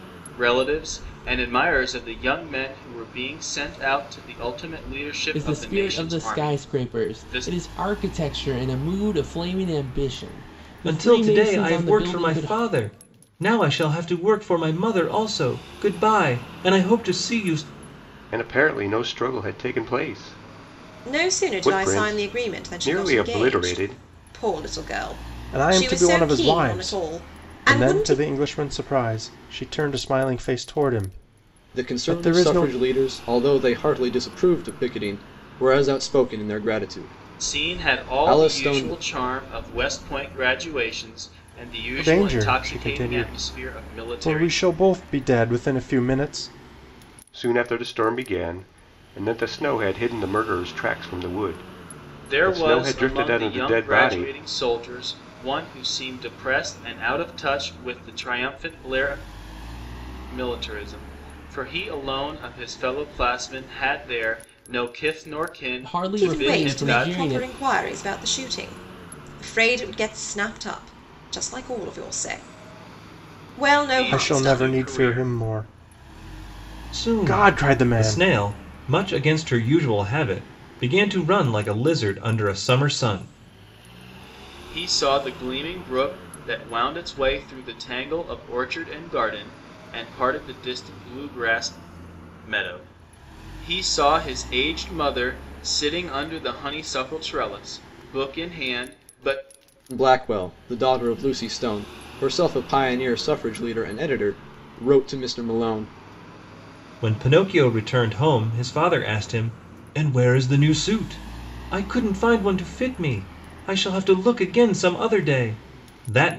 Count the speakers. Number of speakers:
7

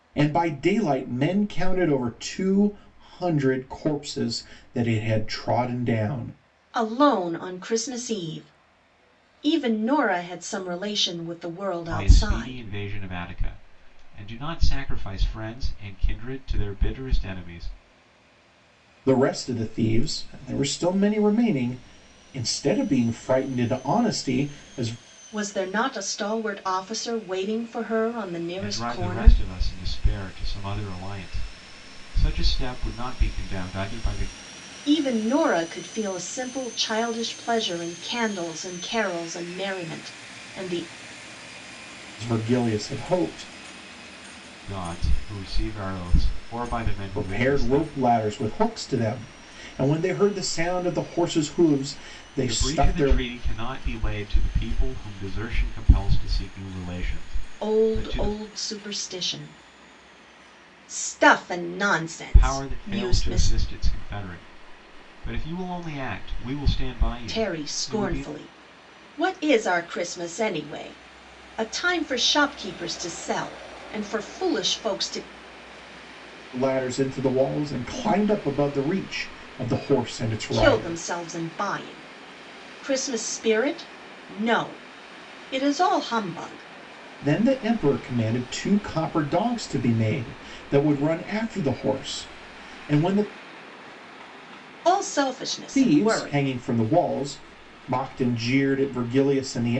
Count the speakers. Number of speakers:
3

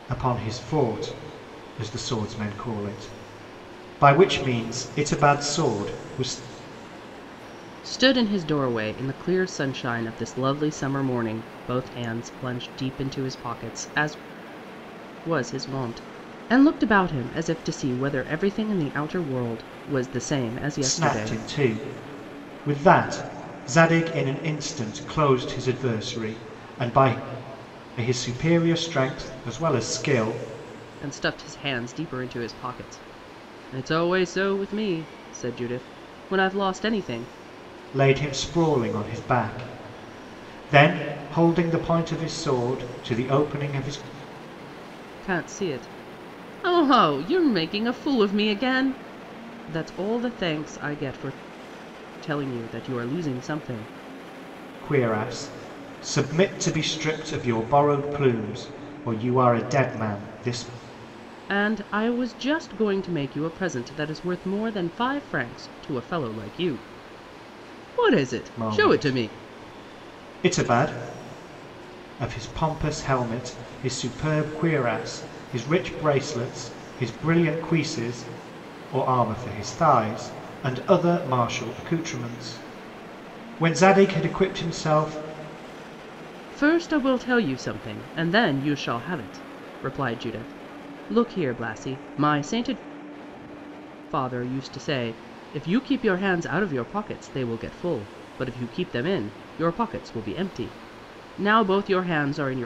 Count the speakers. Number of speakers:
2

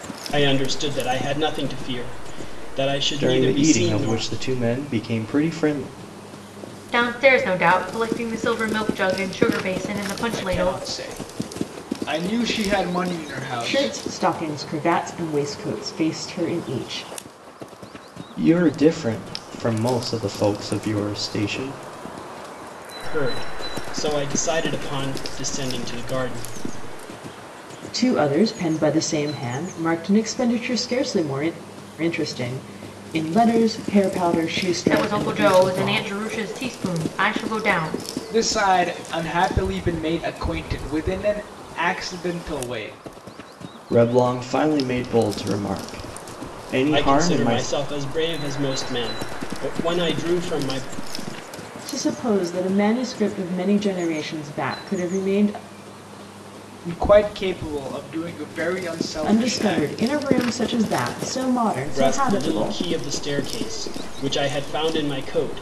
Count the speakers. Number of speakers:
5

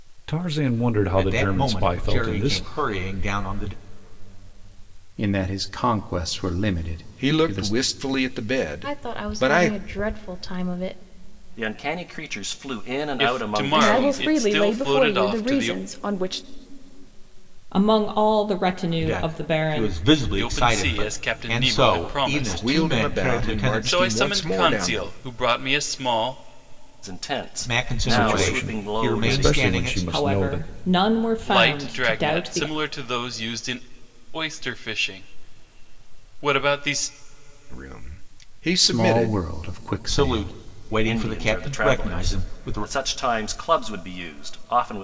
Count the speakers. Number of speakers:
9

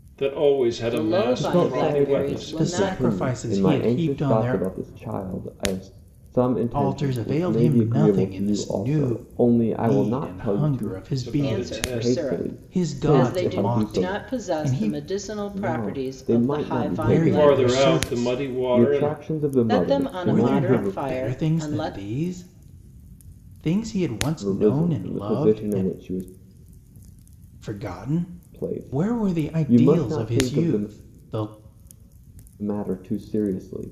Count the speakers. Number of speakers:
4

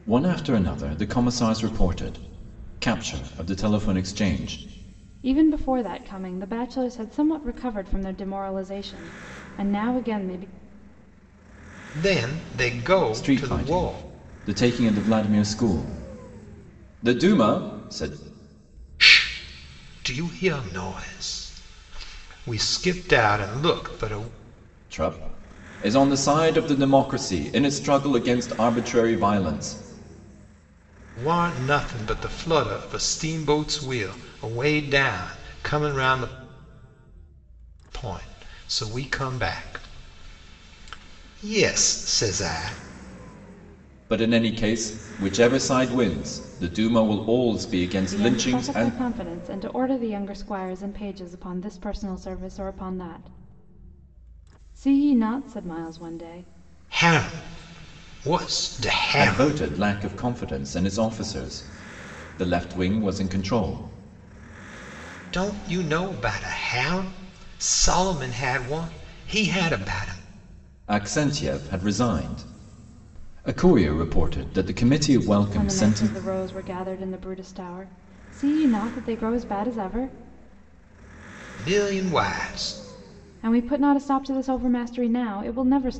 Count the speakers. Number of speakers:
3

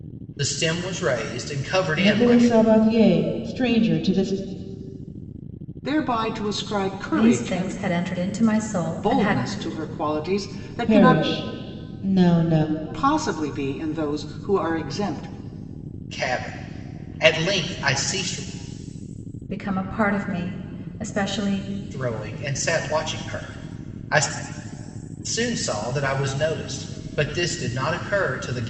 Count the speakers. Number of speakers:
4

